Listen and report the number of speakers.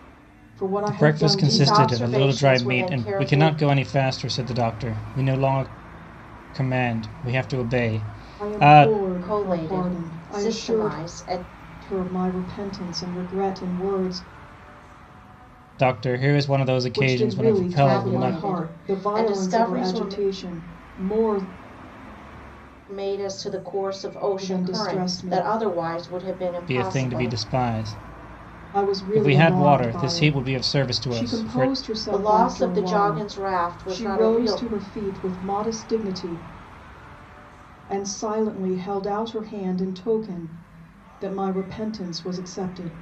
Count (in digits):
3